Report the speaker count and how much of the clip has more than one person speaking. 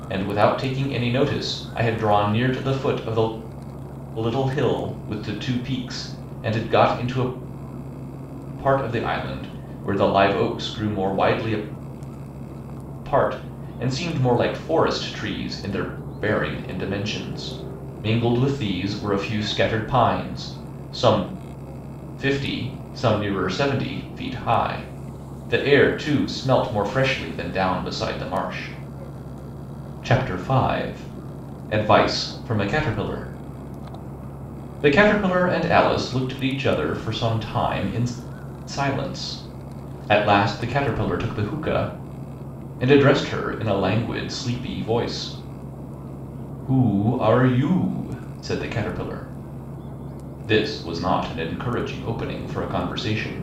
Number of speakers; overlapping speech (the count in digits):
1, no overlap